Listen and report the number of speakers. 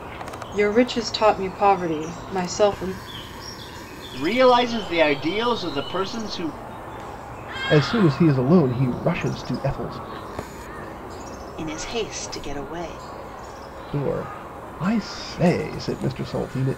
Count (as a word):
four